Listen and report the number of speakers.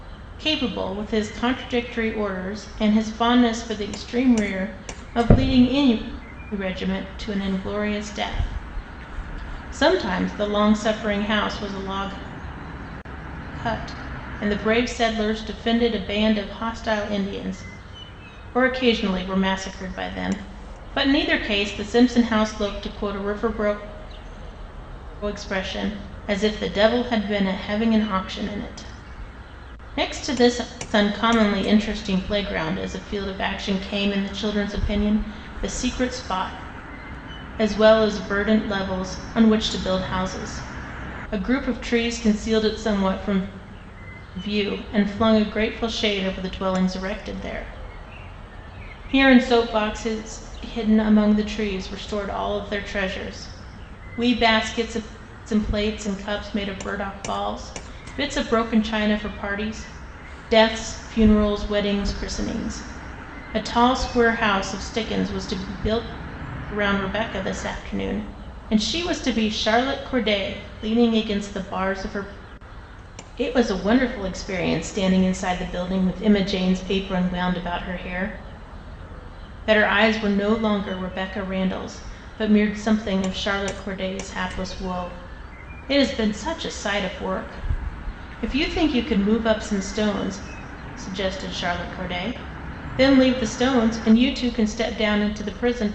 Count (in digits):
1